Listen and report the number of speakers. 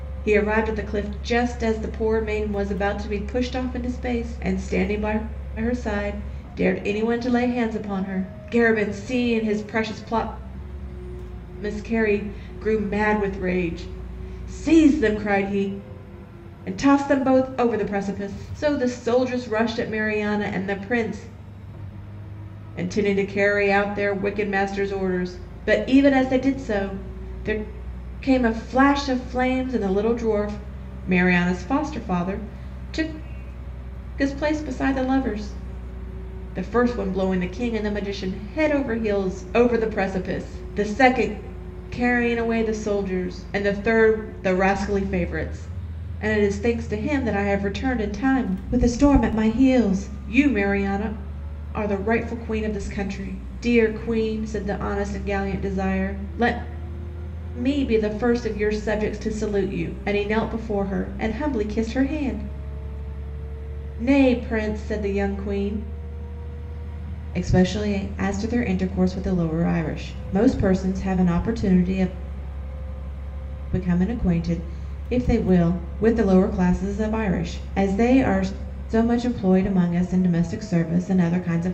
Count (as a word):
one